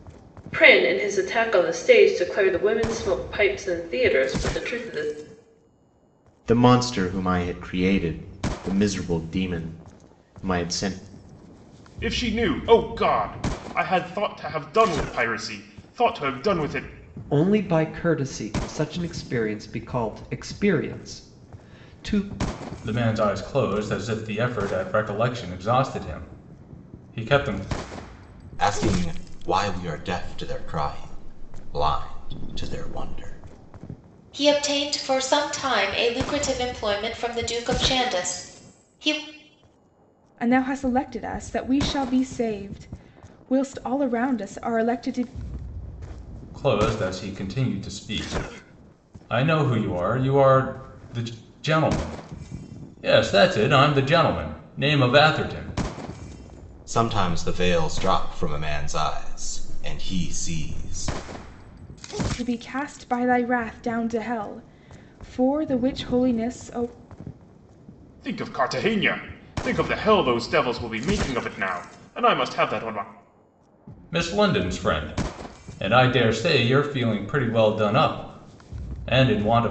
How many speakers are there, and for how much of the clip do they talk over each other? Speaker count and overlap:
eight, no overlap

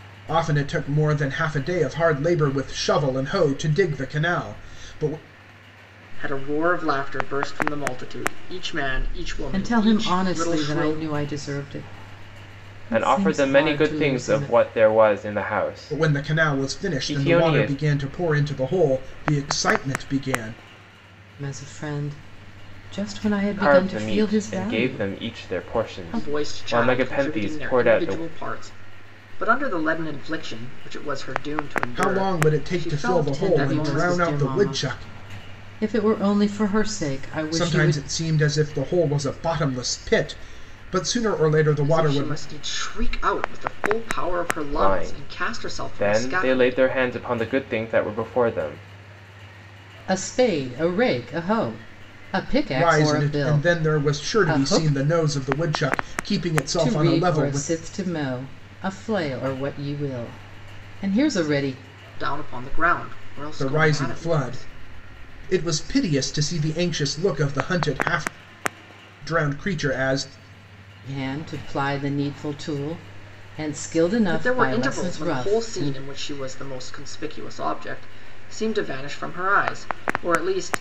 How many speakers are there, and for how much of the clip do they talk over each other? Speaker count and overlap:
four, about 28%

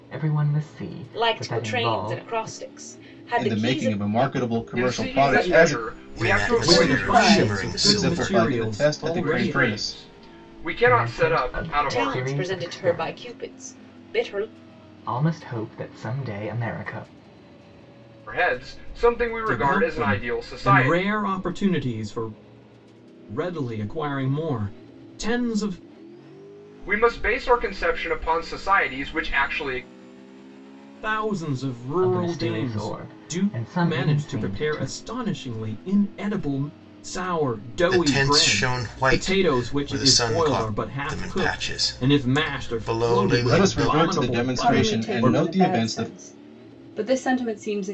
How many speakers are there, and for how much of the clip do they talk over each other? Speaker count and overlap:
seven, about 47%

